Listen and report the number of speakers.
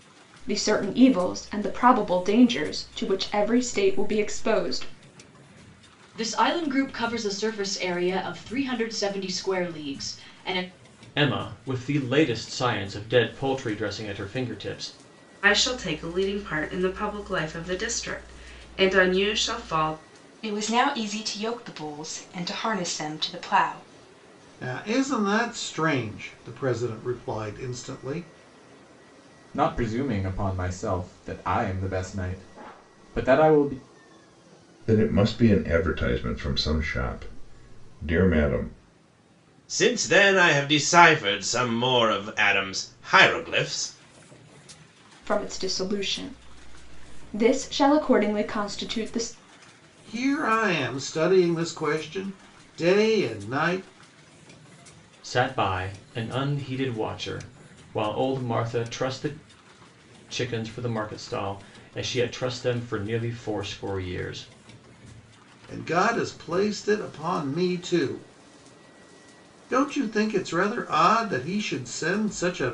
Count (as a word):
nine